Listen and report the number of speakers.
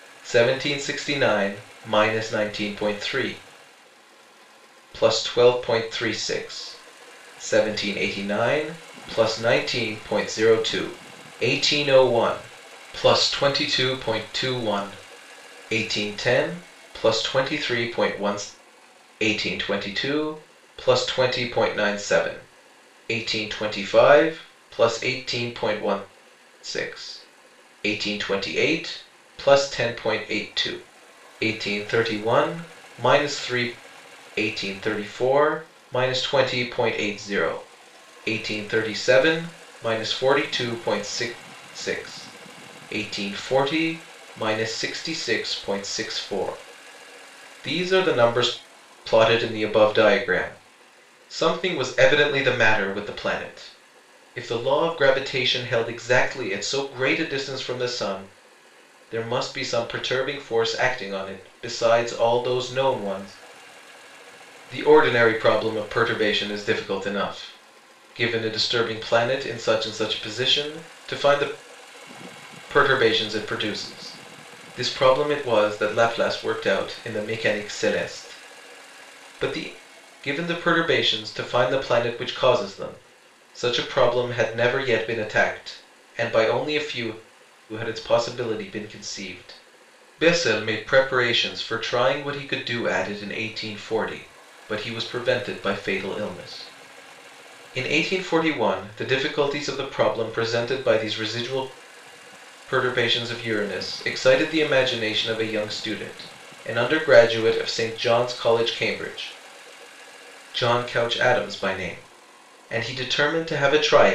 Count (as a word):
one